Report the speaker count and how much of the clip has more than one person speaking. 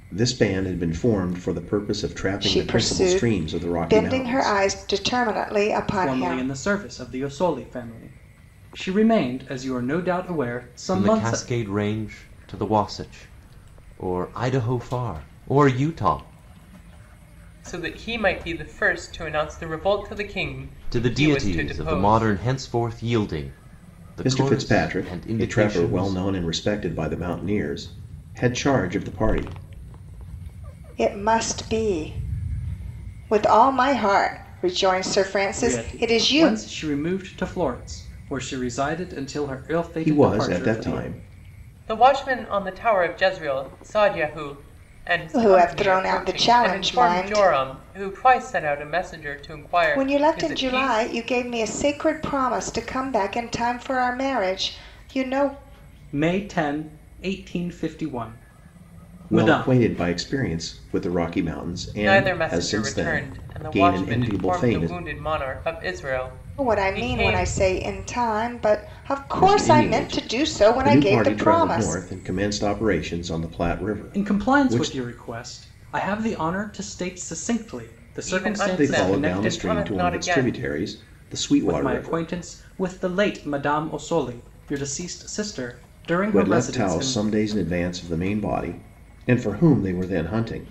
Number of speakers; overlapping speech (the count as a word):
five, about 27%